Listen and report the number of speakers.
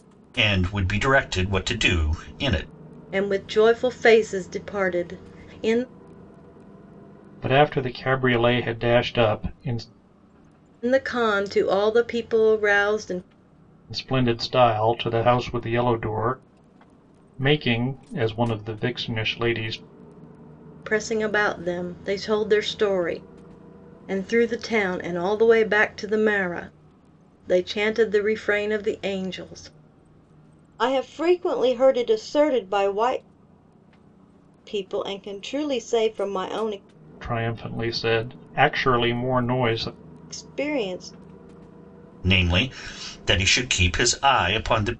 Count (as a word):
three